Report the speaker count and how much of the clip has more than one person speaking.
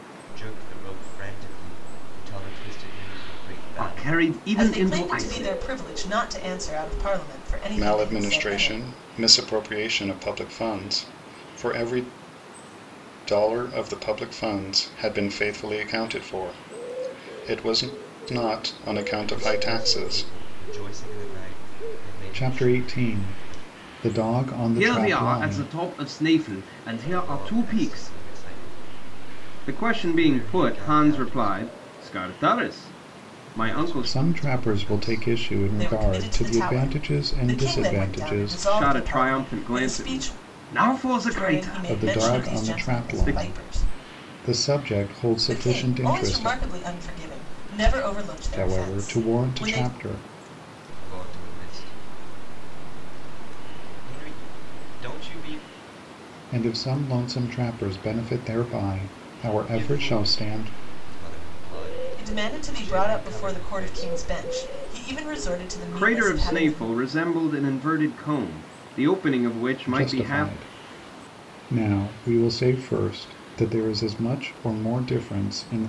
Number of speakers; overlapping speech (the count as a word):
four, about 34%